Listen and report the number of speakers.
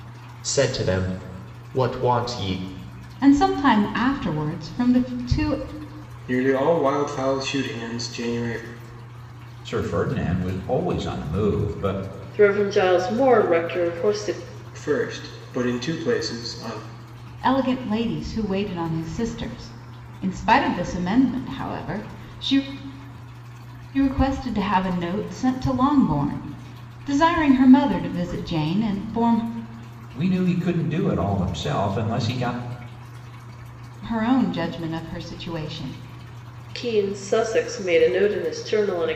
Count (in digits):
5